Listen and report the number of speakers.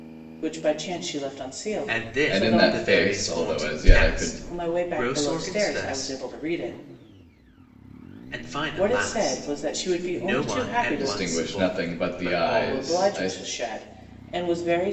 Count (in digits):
3